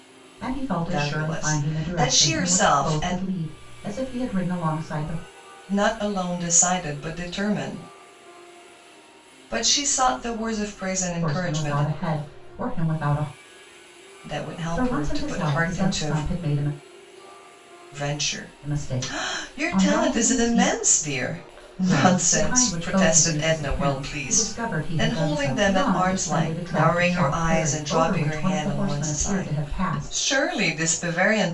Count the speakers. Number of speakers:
2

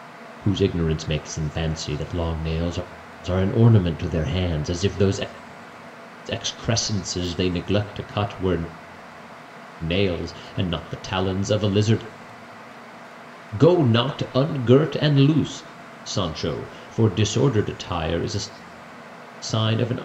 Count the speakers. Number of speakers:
1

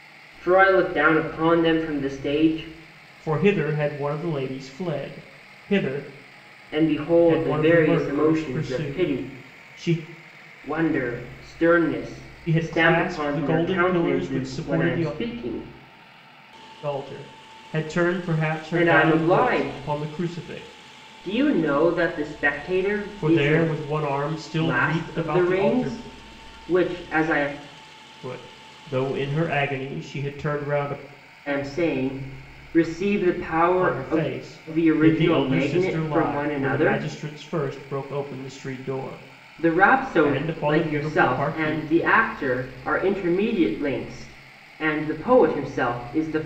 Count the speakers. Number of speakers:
2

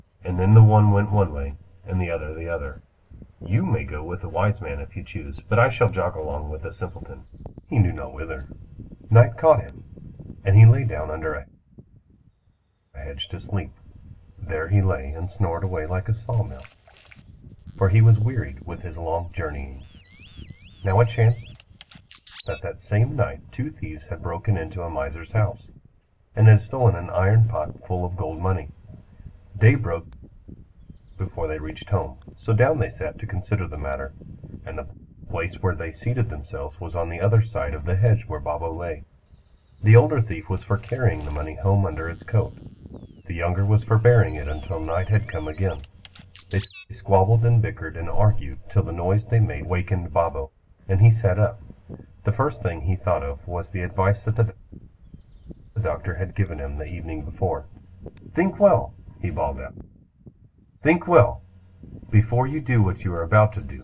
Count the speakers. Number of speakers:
1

